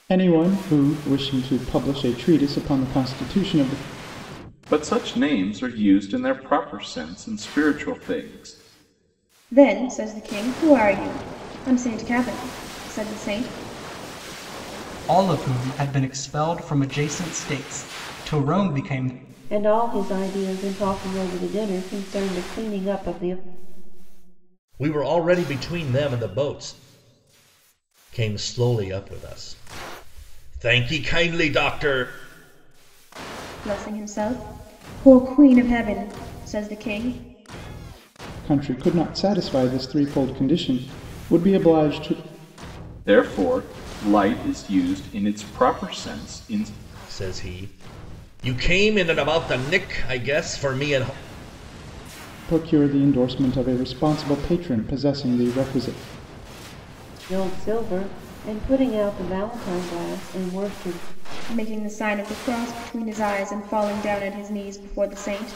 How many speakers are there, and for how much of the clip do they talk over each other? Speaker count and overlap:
six, no overlap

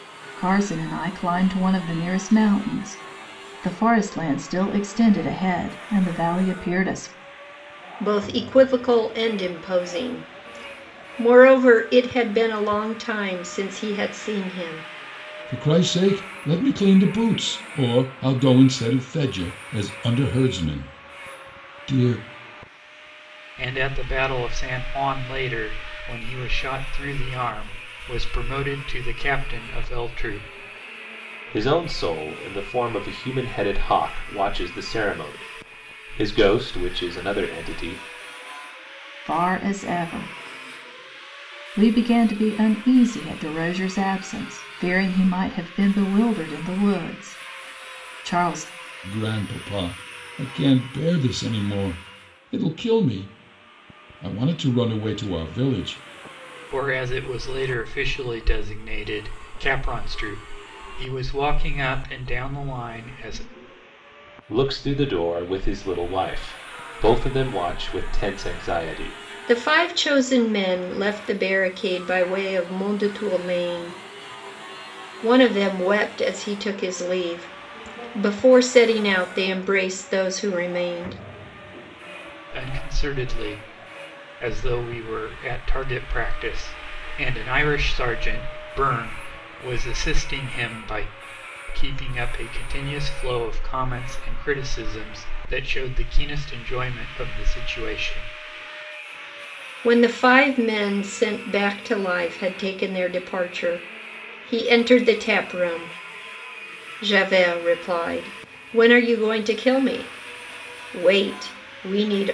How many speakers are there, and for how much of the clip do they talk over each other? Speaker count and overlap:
five, no overlap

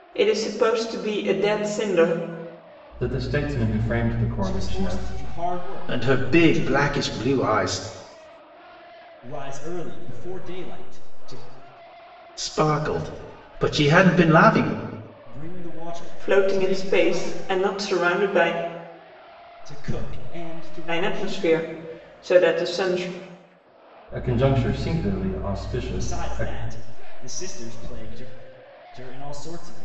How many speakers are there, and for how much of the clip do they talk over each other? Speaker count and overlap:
four, about 13%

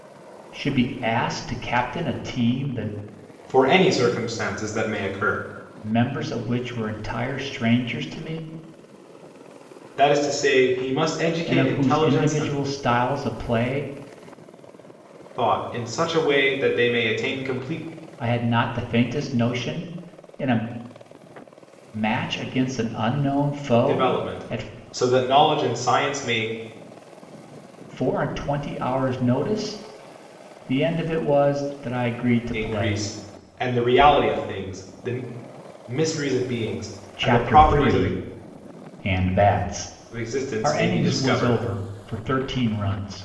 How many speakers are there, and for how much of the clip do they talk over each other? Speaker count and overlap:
two, about 11%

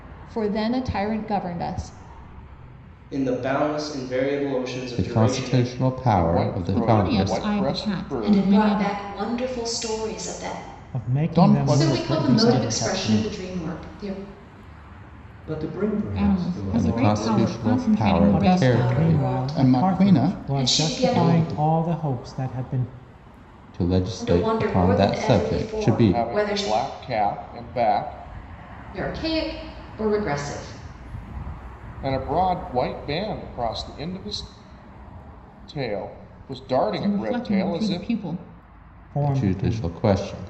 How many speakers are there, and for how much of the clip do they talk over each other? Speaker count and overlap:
ten, about 38%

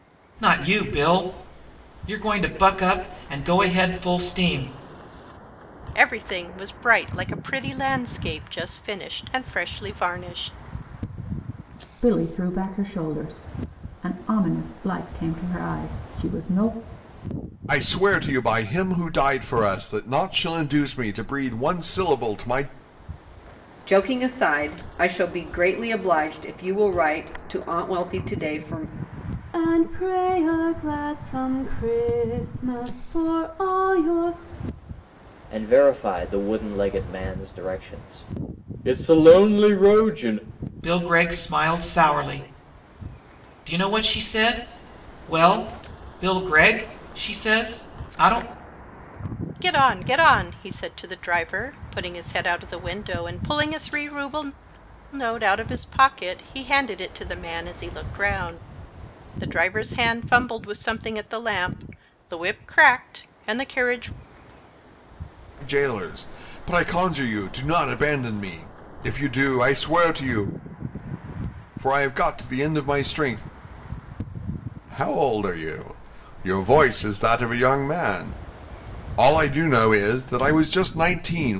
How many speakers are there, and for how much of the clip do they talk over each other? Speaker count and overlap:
seven, no overlap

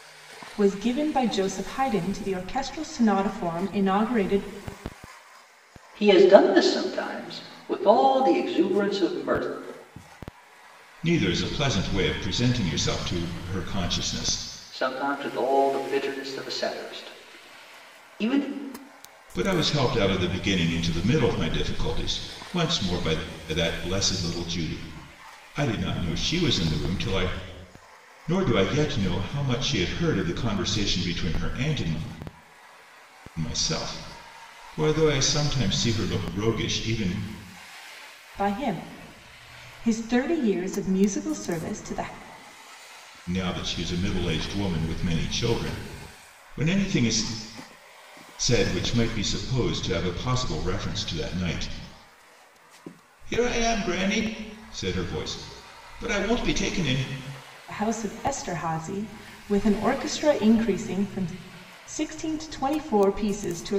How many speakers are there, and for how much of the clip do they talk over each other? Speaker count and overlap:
three, no overlap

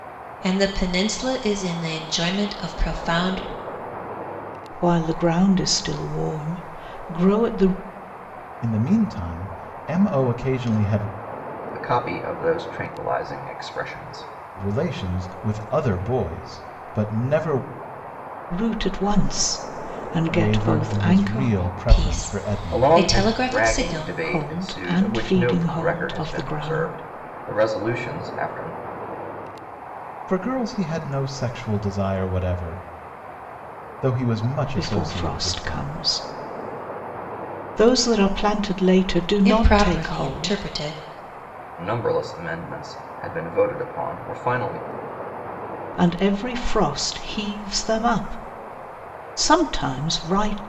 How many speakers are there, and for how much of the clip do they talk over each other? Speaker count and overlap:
four, about 17%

